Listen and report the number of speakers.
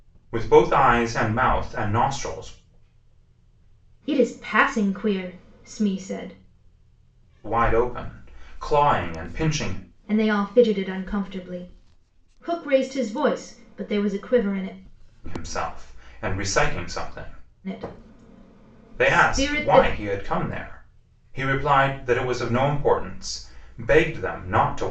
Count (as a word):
two